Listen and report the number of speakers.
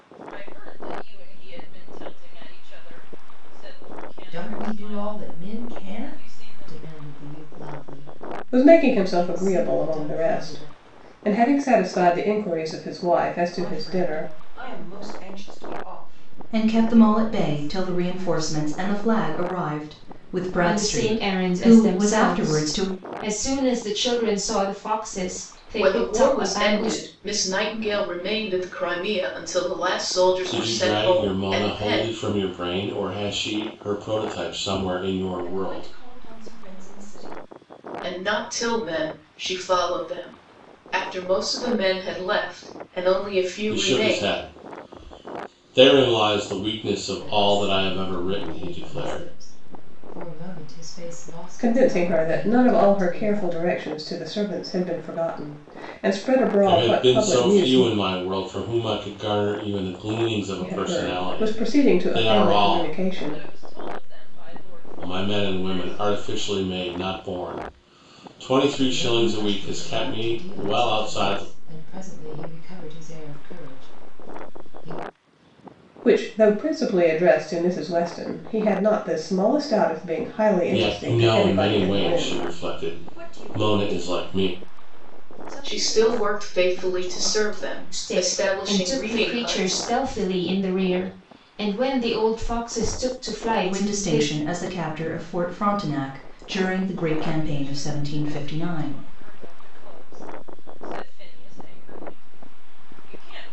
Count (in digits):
8